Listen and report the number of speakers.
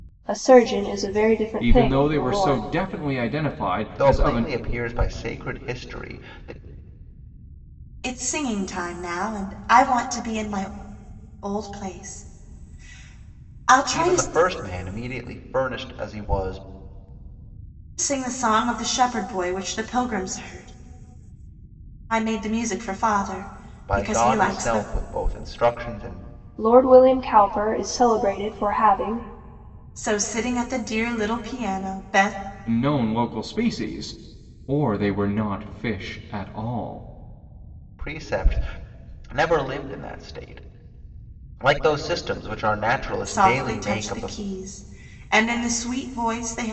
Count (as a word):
four